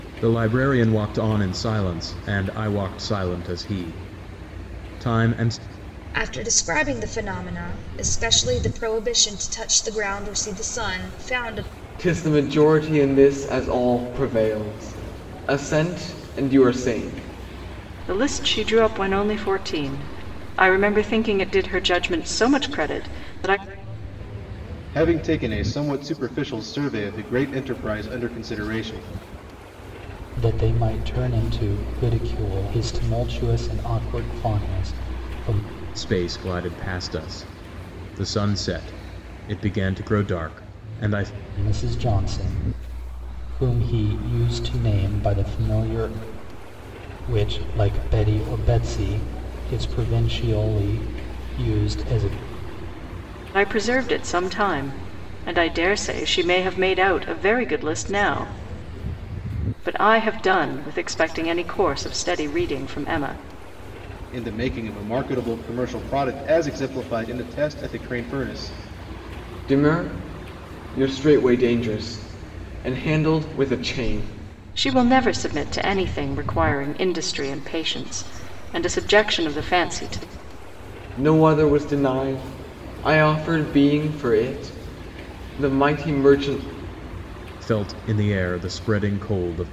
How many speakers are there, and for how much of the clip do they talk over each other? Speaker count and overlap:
six, no overlap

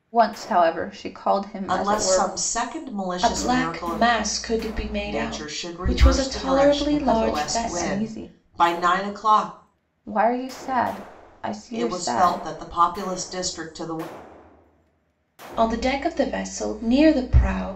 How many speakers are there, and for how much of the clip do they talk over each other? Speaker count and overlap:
three, about 30%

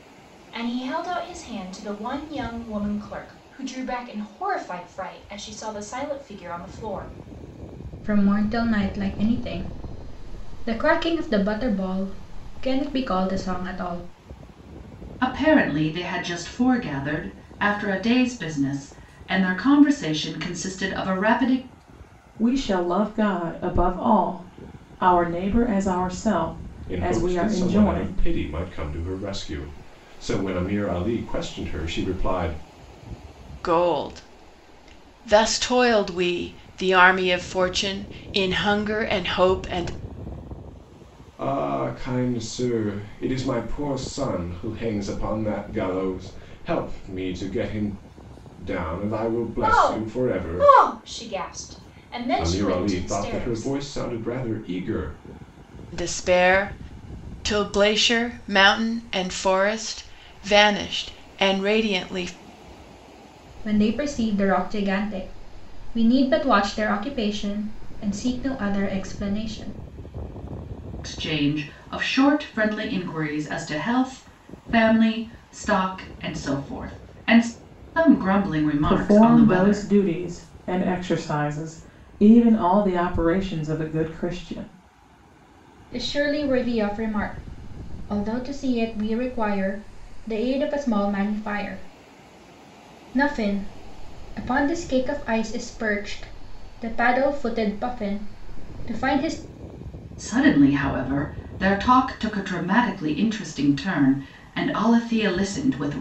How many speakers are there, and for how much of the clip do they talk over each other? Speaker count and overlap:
six, about 5%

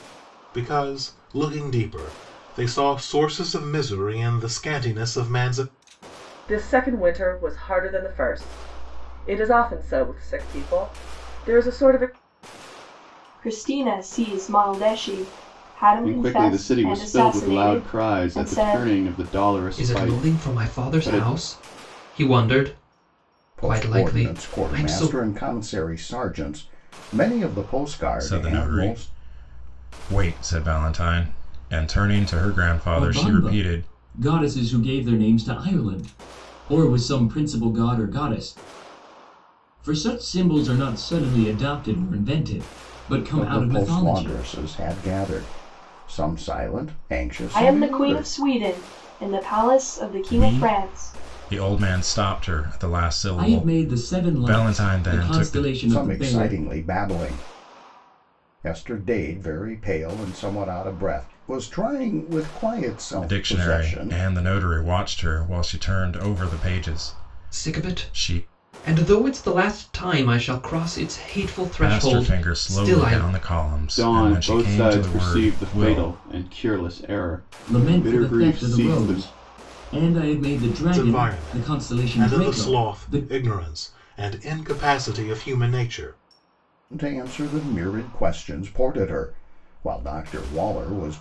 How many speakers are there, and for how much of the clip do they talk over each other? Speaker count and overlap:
eight, about 26%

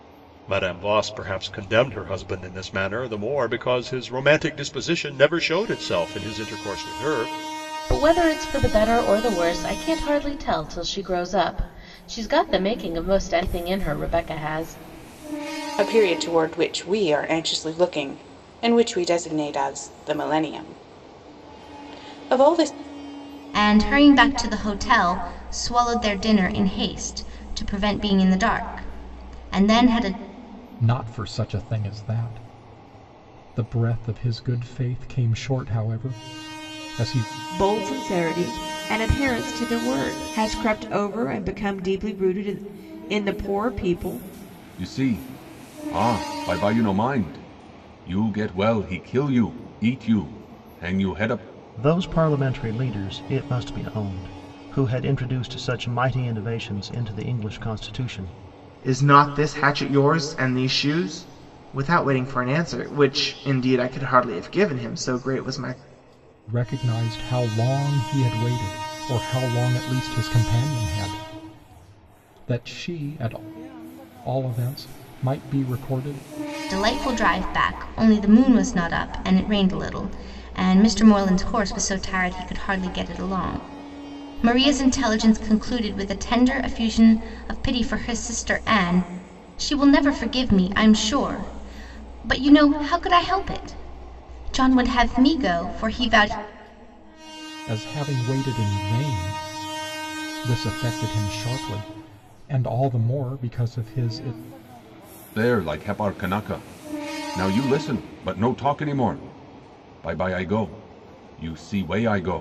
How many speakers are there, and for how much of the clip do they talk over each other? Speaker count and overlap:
nine, no overlap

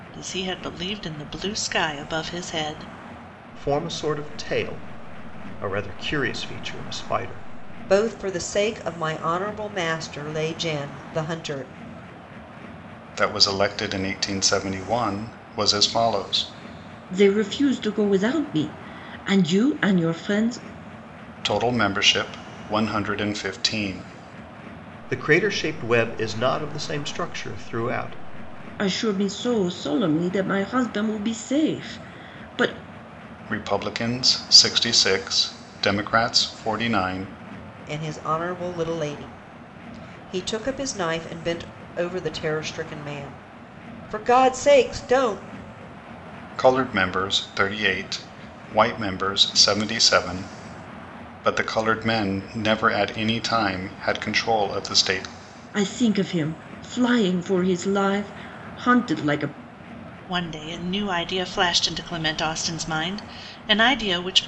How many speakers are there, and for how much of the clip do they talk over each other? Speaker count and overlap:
five, no overlap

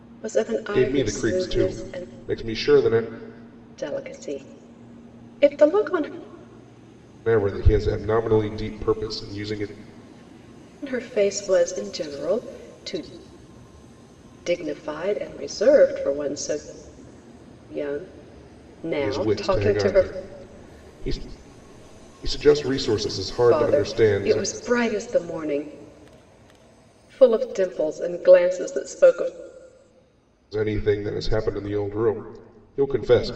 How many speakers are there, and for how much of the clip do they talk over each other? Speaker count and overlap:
two, about 11%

